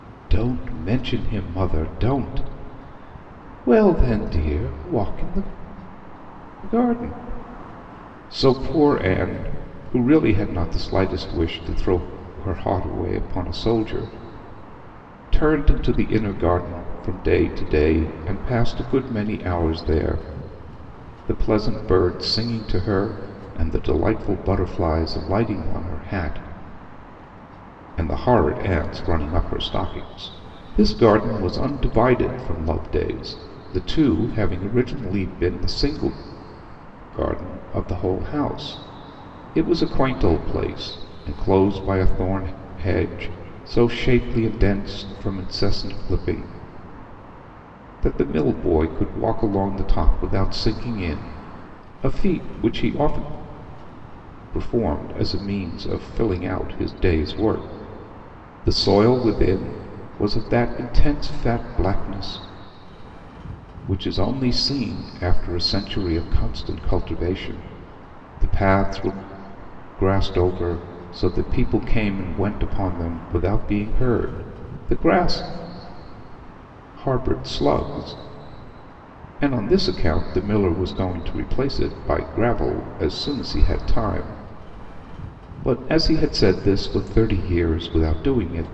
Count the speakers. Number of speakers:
one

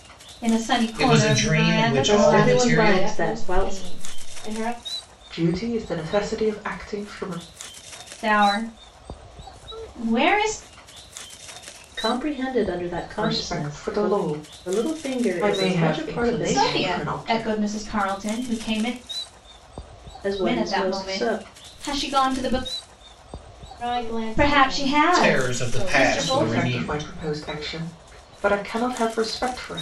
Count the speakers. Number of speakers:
five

